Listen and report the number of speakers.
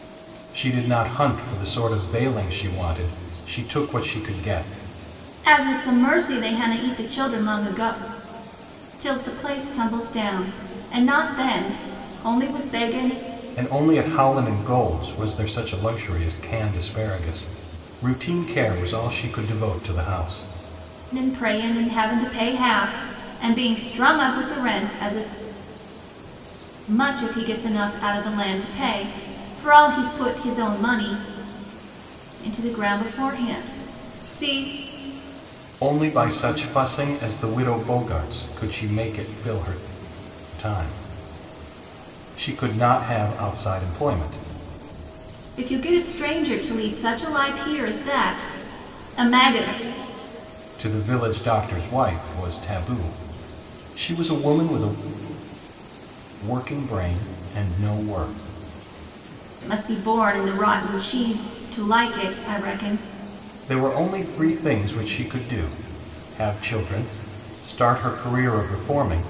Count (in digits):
2